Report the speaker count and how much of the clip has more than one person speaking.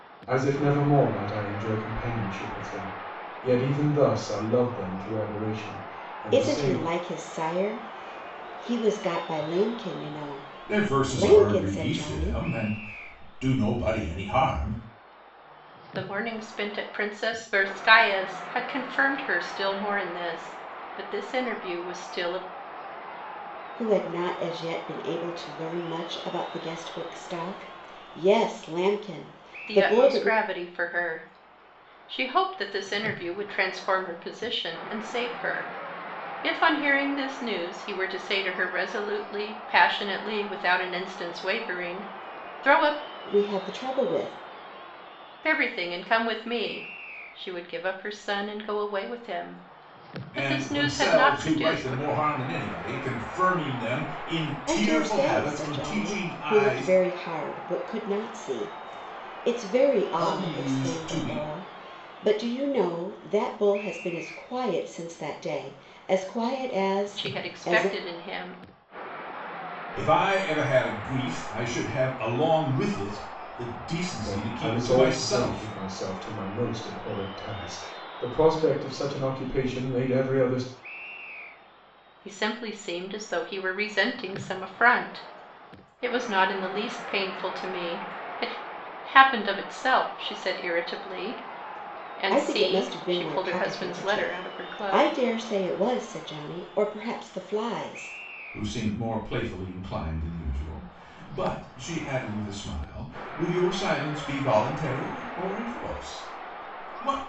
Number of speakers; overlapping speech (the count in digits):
4, about 13%